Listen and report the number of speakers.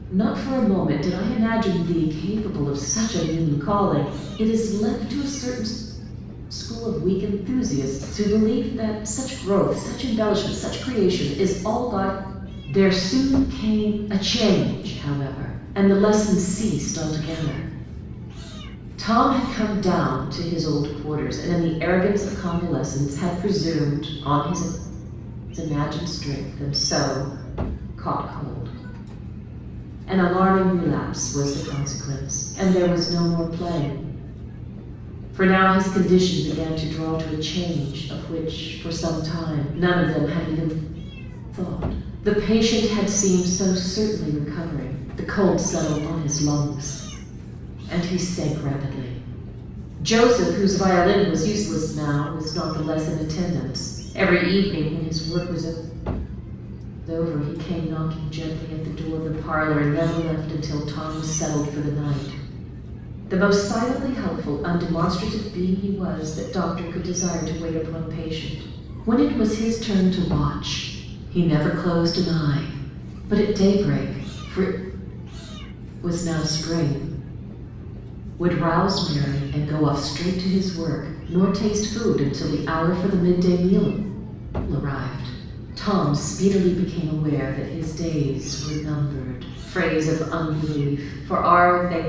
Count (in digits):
1